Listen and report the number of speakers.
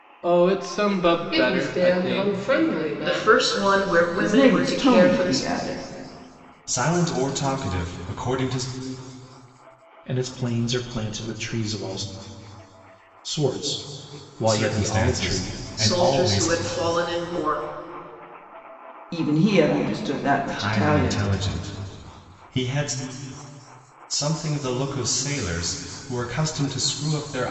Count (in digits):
6